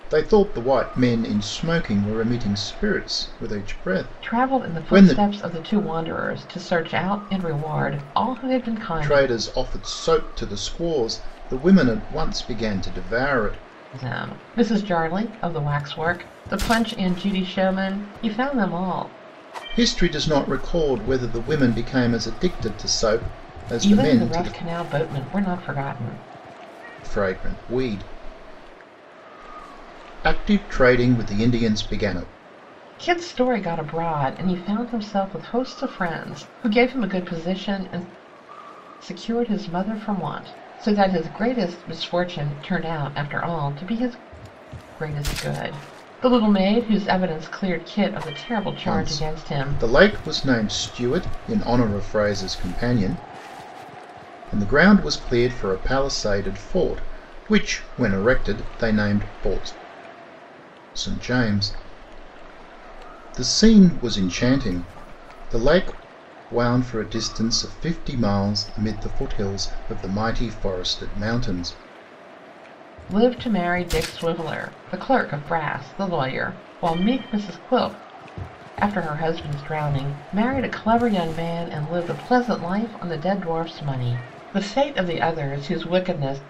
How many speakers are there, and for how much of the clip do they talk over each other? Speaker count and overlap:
2, about 4%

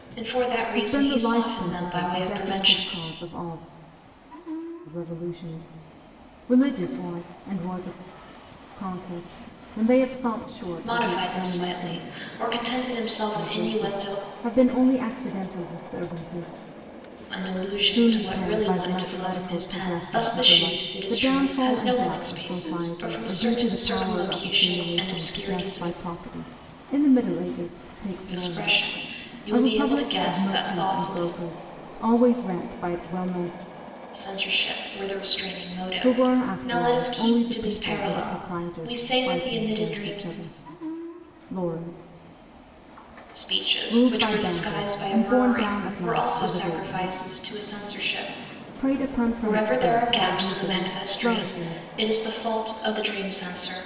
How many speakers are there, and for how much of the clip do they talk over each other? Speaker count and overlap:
2, about 47%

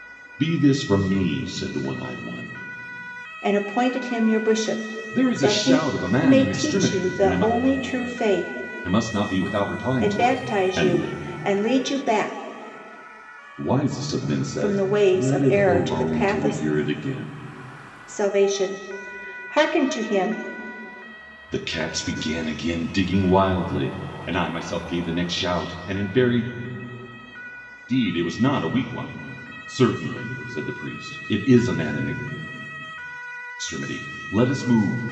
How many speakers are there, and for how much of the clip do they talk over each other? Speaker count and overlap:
2, about 15%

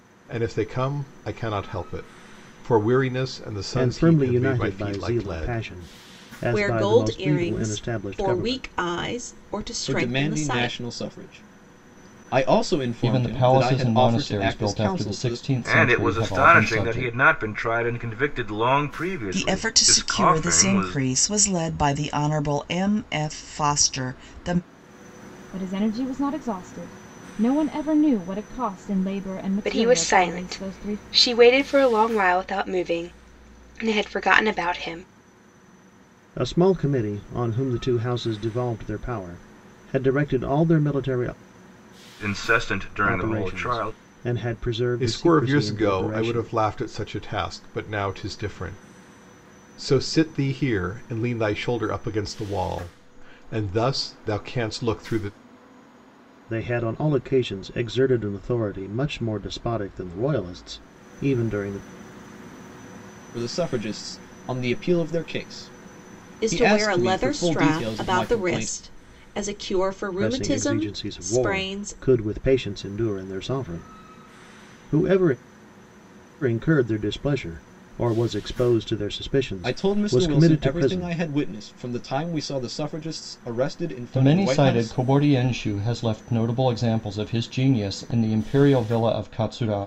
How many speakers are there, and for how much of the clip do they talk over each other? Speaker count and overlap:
9, about 24%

